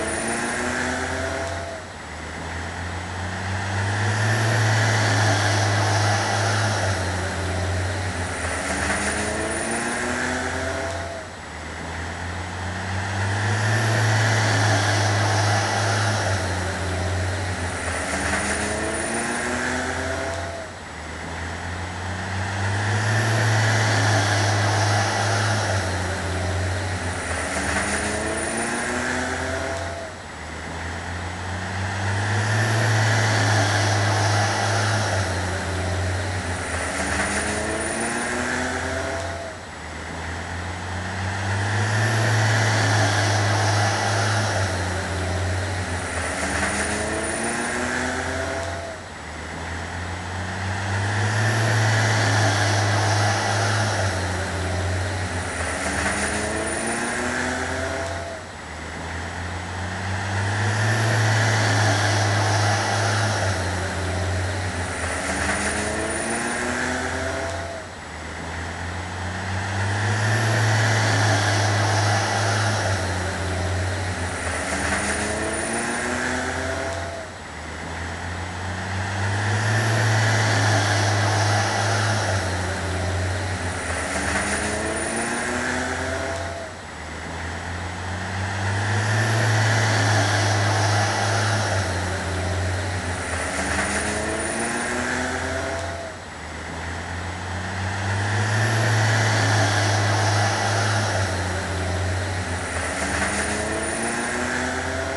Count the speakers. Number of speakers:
0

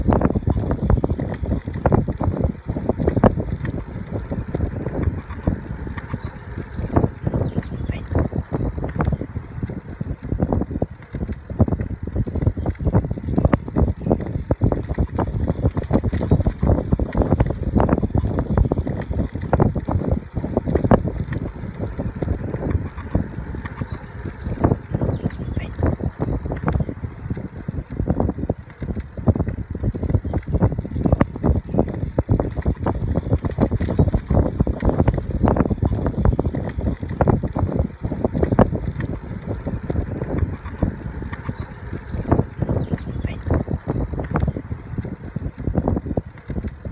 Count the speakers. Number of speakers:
0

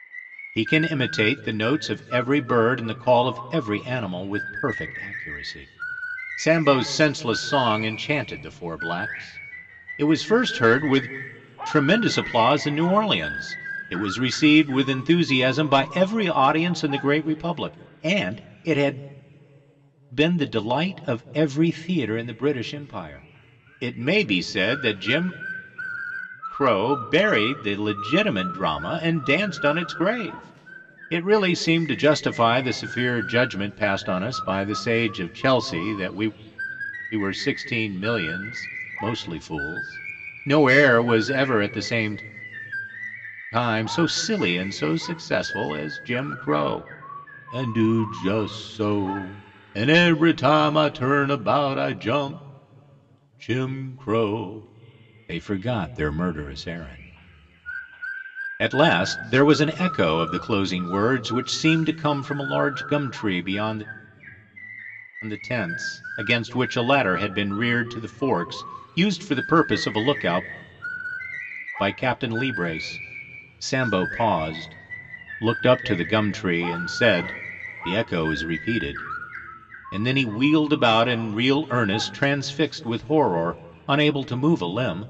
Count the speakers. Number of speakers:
1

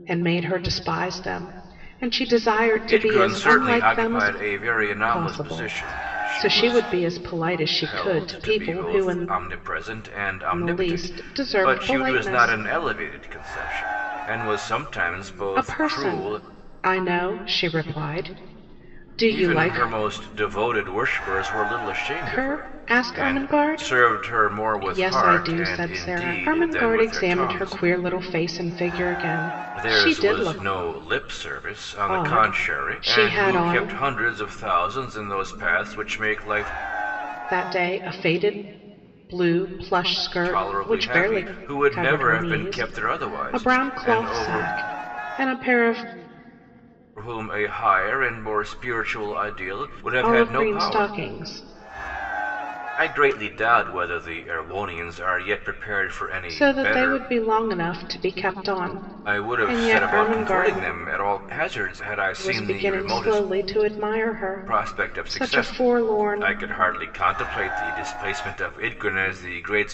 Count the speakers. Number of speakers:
2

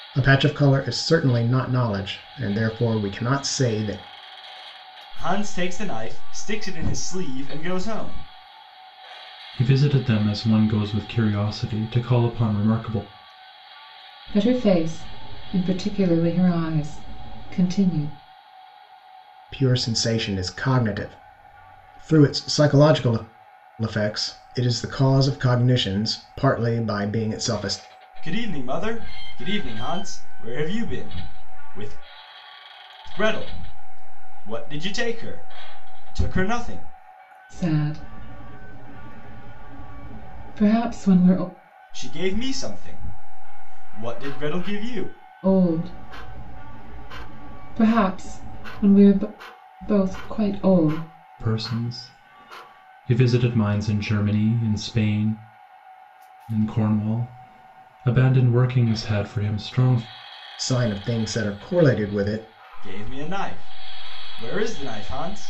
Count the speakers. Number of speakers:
4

